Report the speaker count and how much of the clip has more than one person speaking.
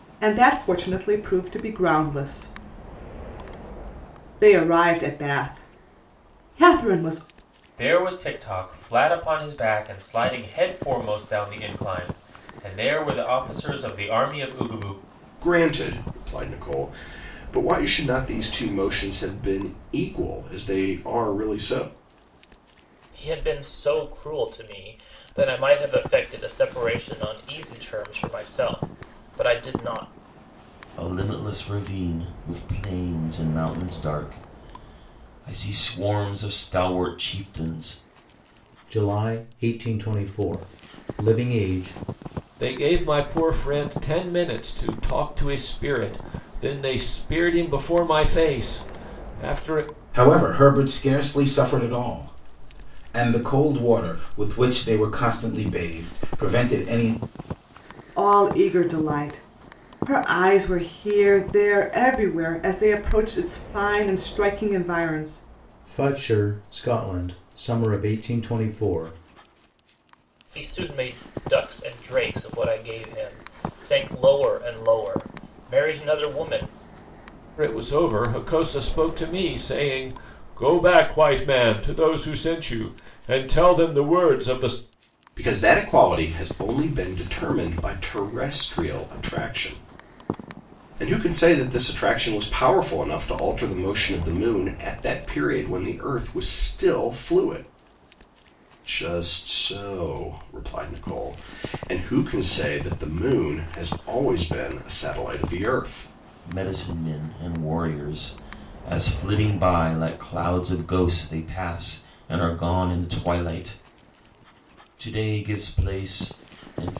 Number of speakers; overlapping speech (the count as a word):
eight, no overlap